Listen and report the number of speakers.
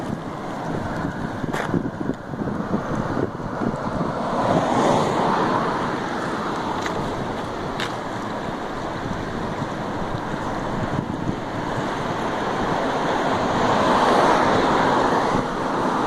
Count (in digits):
0